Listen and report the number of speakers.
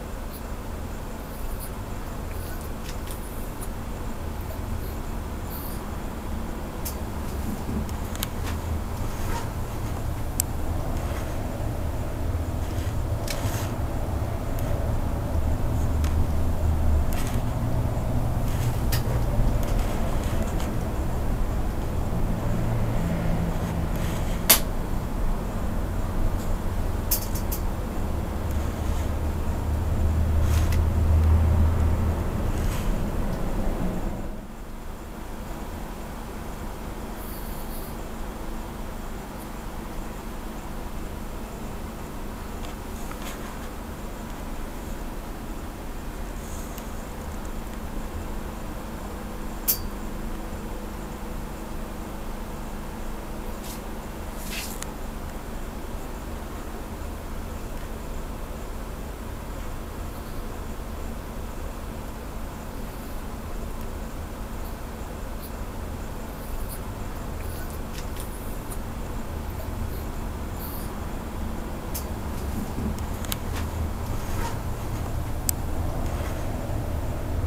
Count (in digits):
0